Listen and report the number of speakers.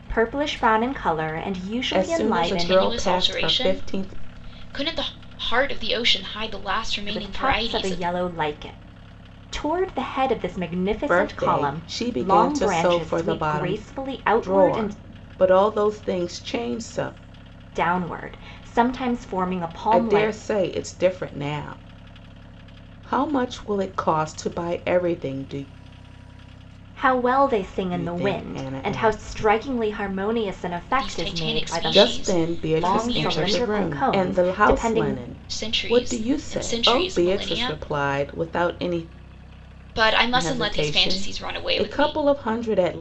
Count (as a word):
three